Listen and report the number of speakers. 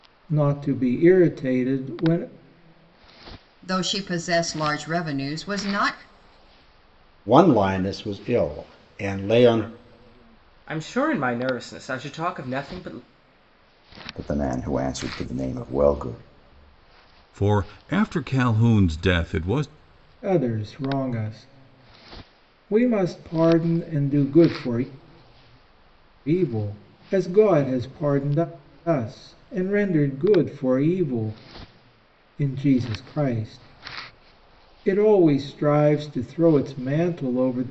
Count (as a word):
six